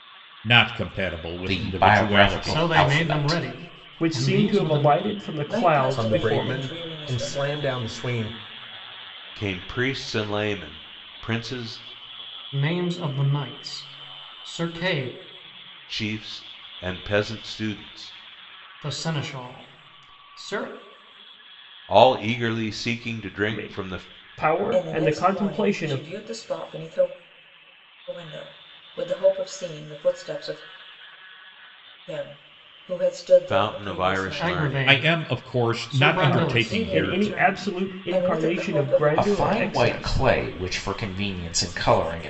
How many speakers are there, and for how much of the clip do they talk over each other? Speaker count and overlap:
seven, about 33%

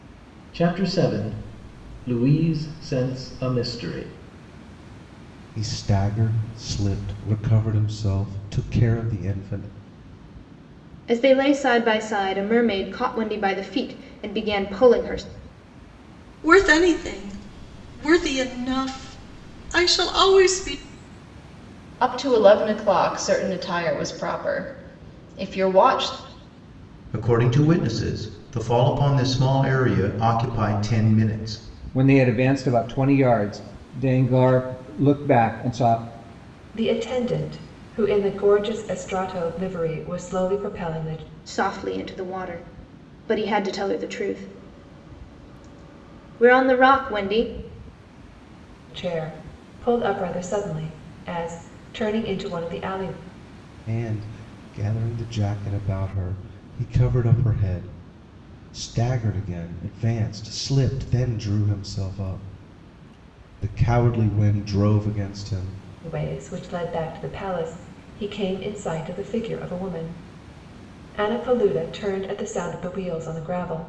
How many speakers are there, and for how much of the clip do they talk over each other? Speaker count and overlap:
eight, no overlap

